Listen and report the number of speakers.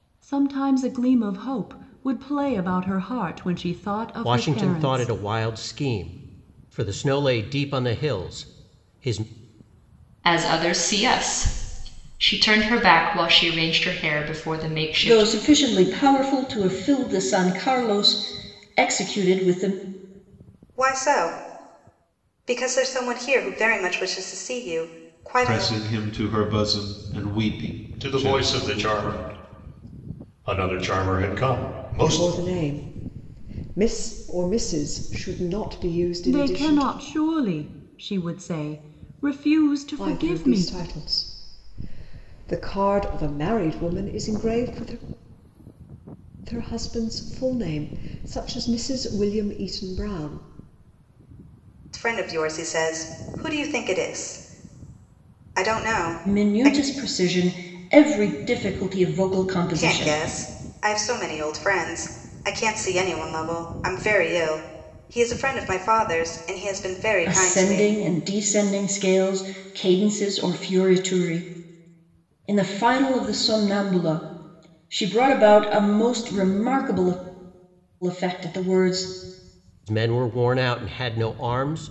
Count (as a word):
eight